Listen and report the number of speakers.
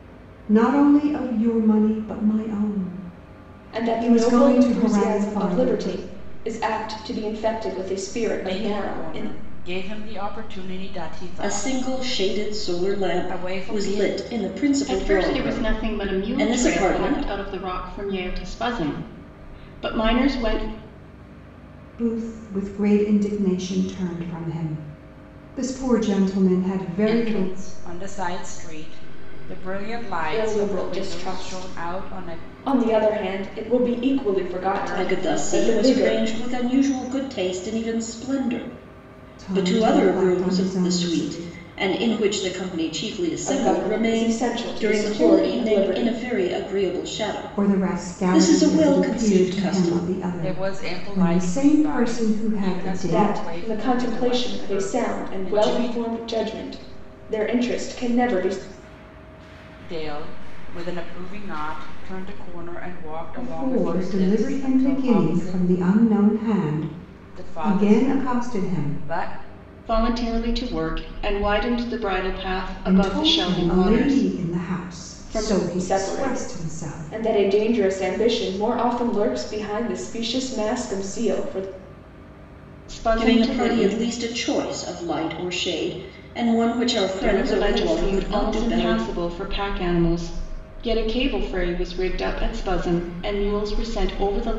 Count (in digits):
5